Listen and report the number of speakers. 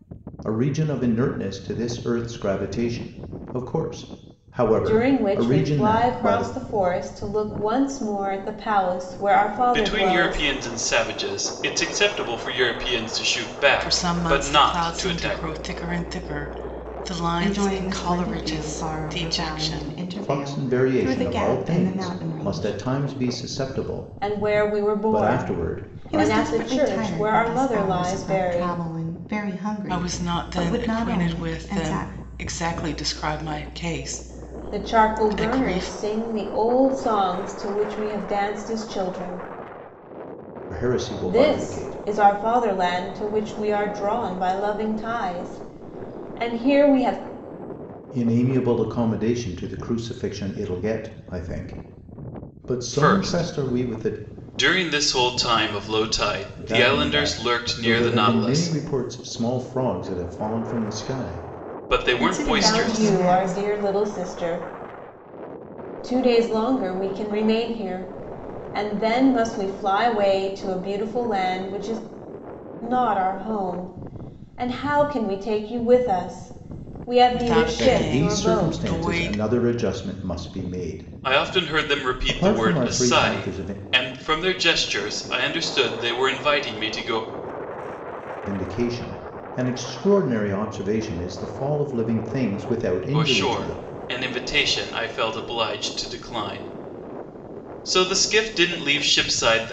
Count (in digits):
5